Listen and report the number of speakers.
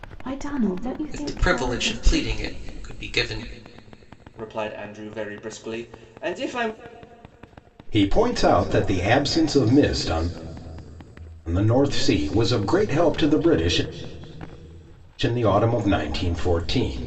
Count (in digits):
4